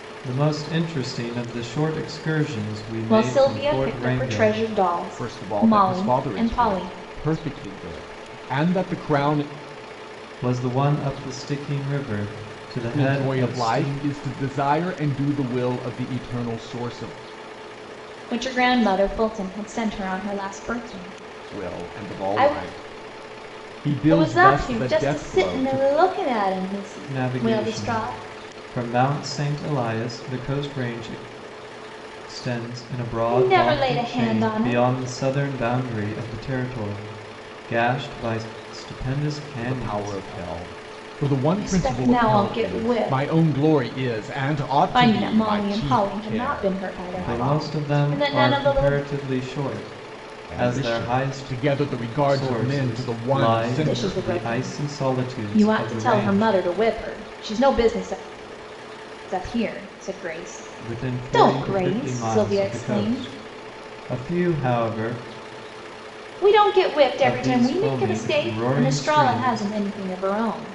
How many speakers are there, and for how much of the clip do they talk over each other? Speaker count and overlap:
three, about 38%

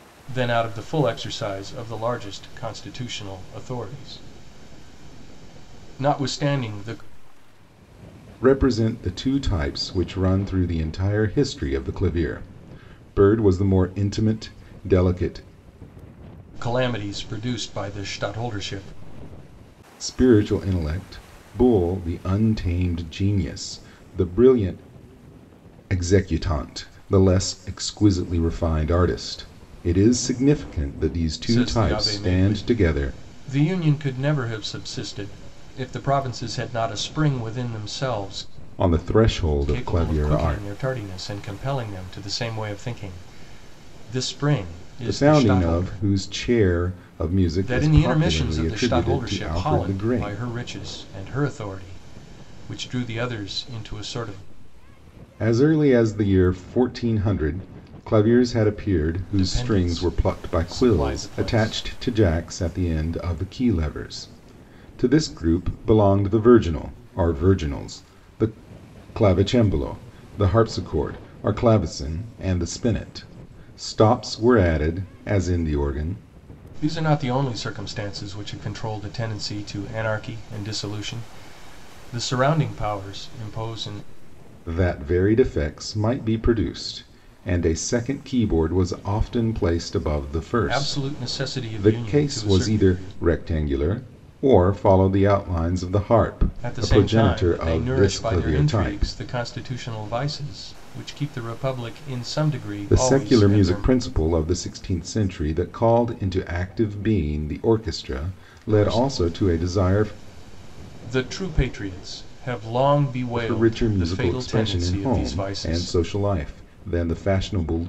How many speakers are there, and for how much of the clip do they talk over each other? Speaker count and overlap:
two, about 16%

